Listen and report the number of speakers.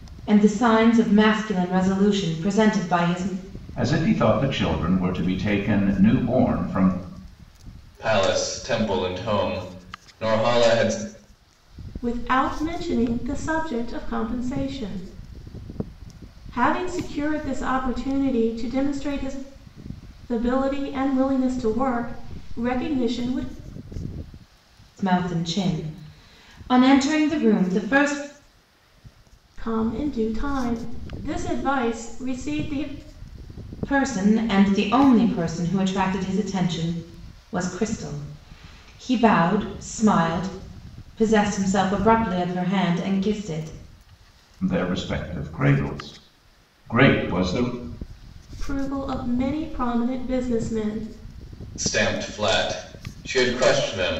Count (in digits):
4